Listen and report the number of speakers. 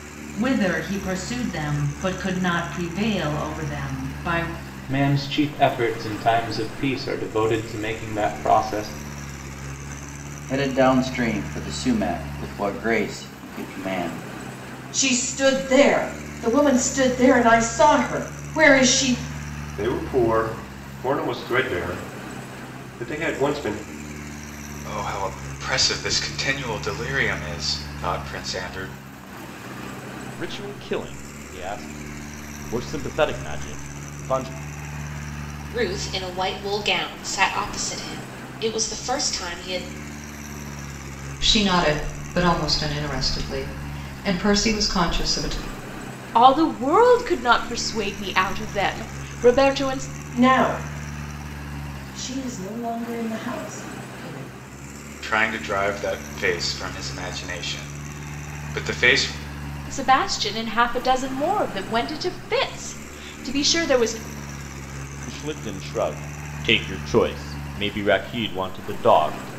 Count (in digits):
10